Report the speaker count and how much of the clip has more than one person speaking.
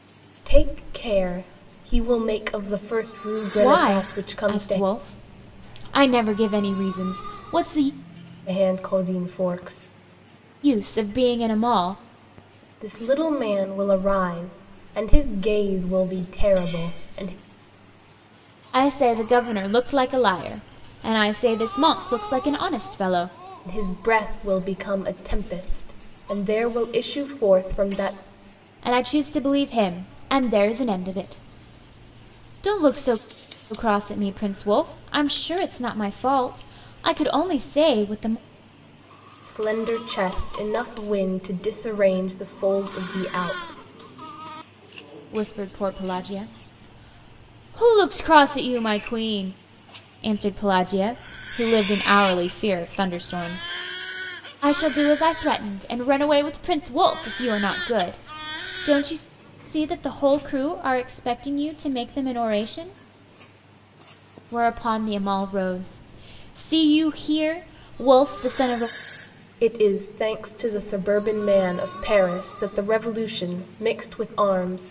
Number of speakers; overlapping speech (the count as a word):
two, about 2%